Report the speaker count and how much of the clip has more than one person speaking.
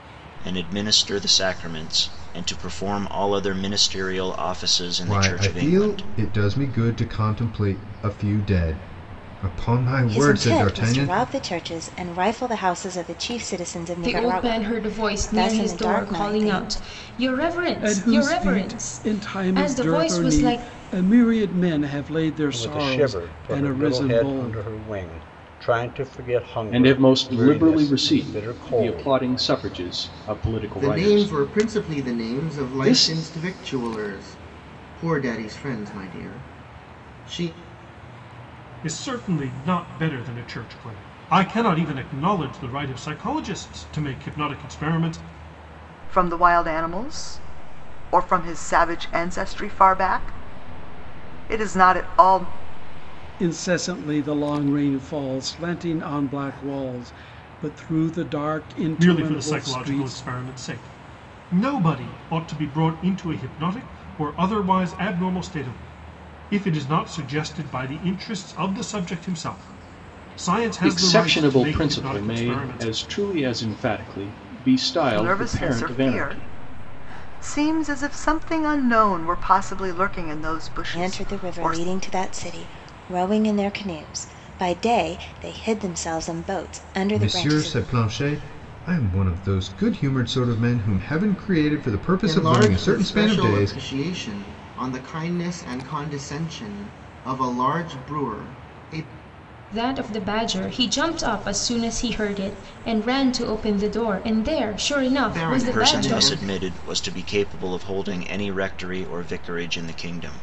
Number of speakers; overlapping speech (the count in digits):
10, about 22%